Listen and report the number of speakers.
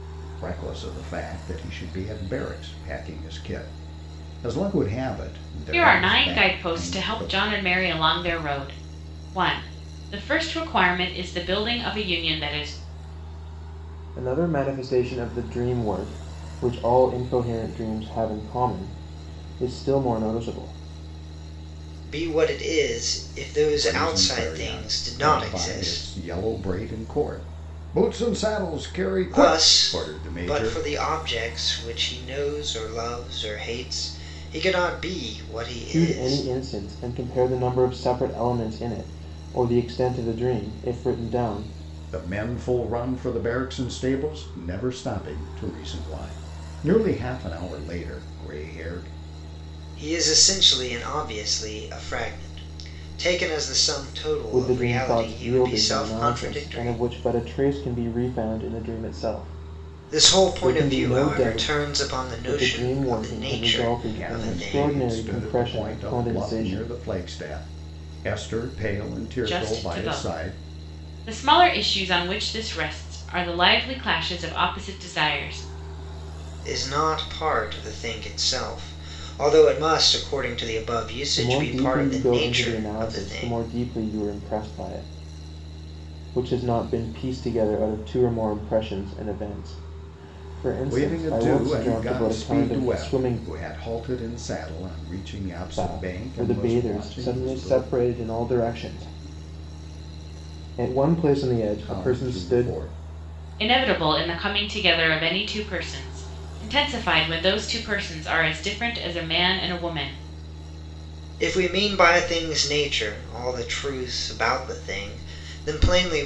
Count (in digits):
4